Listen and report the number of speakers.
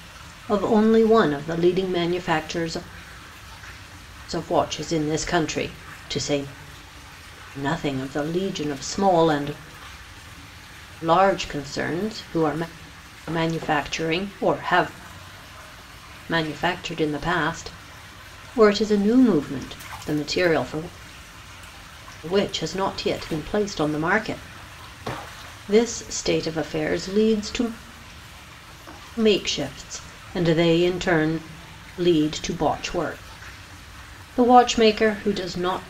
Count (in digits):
1